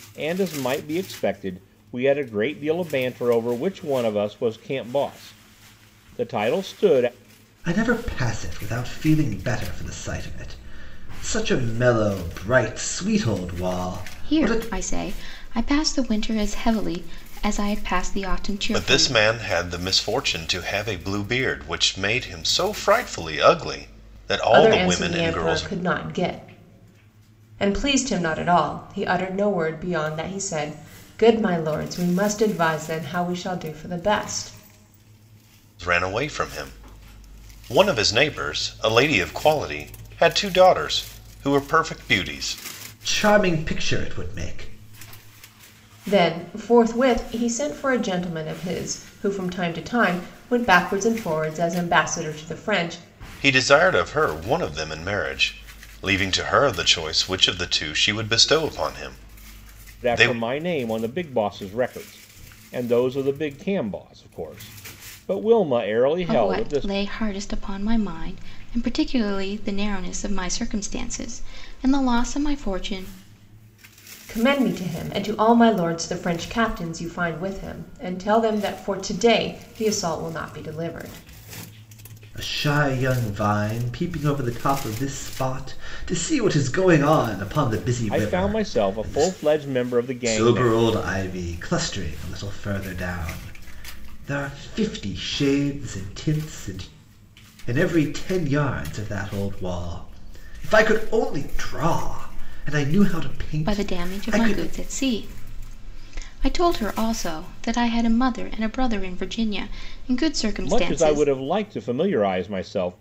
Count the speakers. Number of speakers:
5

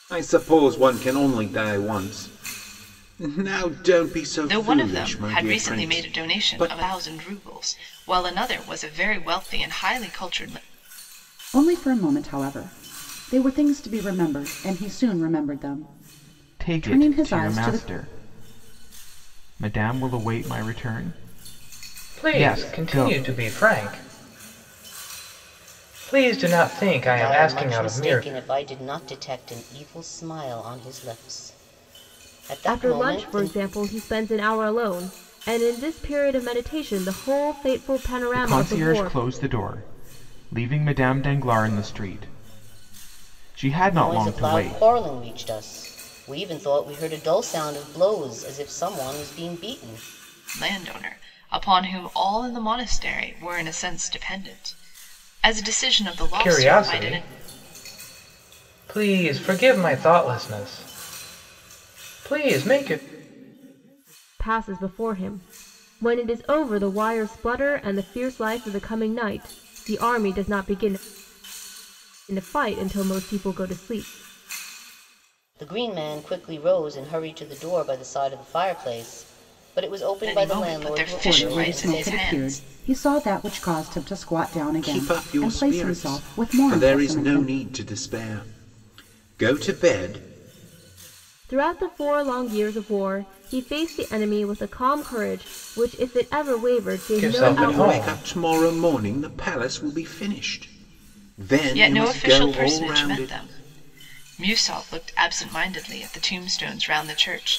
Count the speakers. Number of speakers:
7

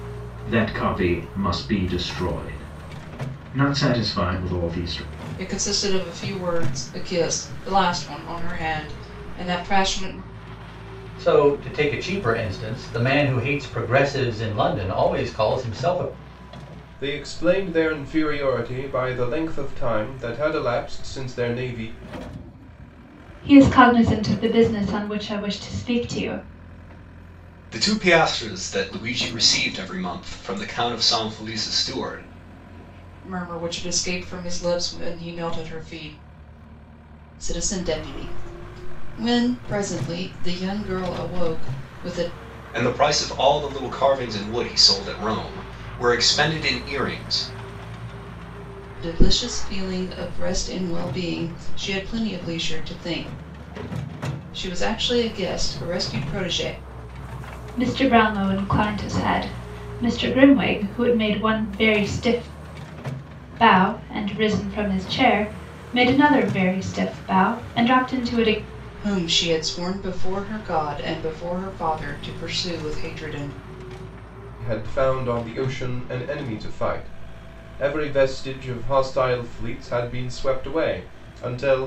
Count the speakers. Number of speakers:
6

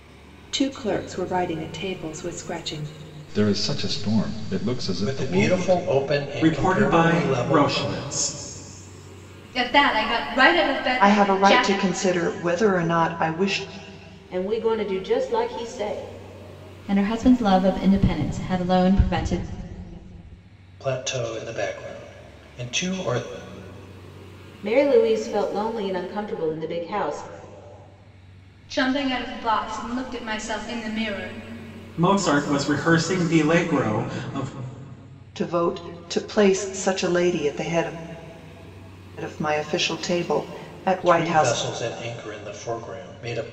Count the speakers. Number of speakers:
8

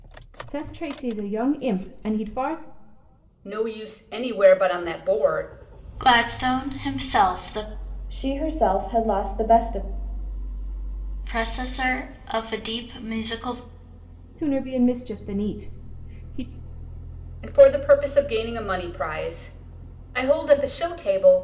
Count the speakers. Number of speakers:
4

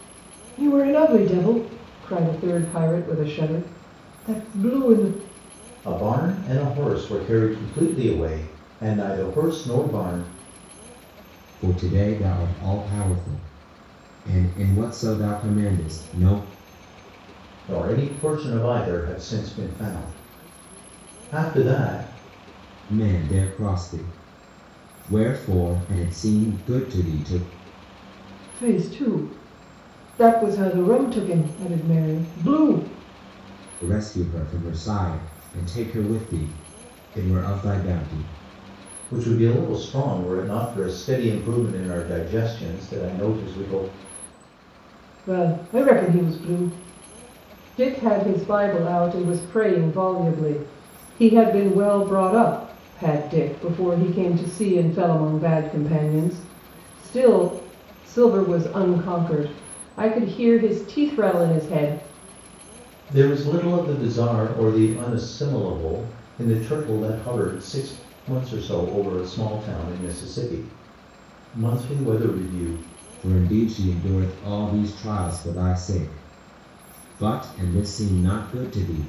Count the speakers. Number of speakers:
3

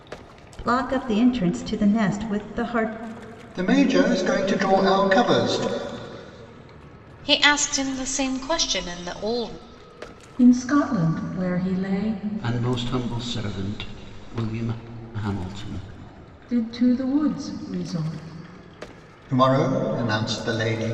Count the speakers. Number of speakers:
5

